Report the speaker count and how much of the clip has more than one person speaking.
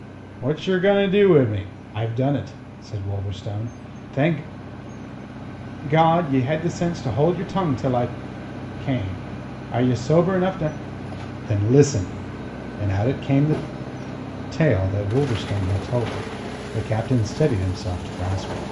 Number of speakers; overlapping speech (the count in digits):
1, no overlap